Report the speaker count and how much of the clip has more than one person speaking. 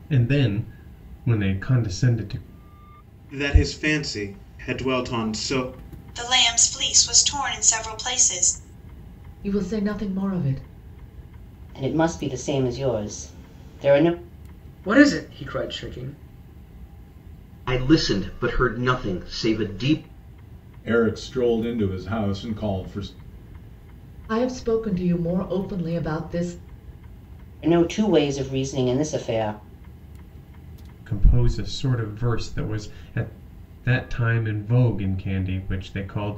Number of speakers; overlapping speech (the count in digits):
8, no overlap